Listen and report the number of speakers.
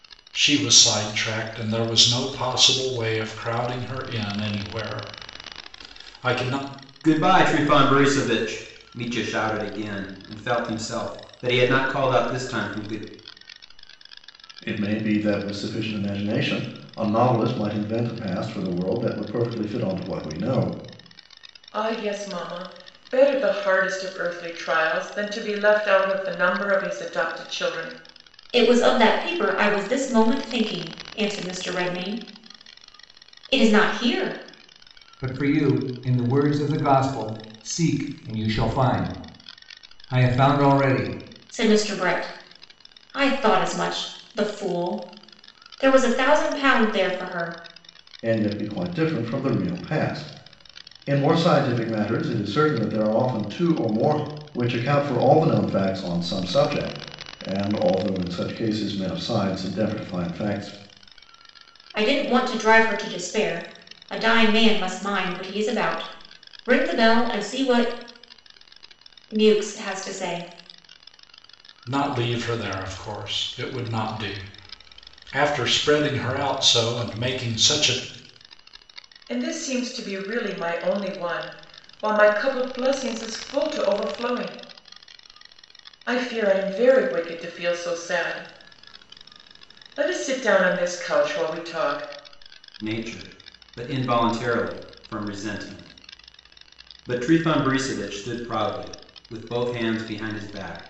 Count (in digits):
6